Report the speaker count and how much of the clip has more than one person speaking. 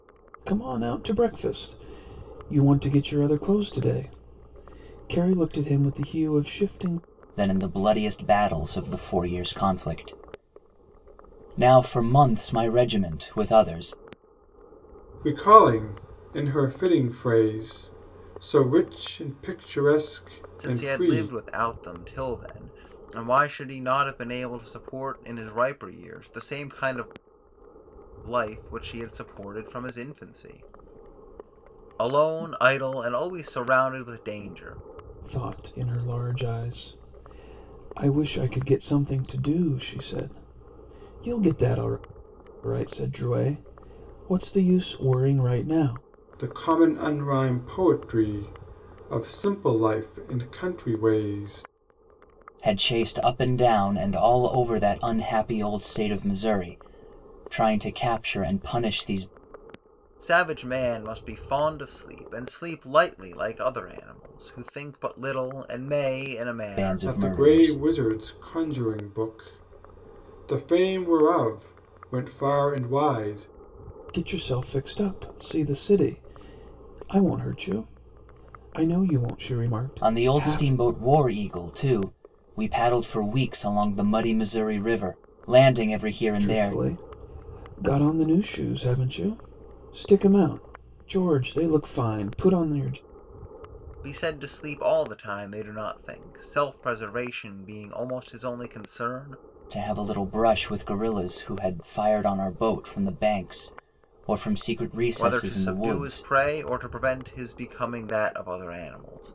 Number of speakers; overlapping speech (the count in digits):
4, about 4%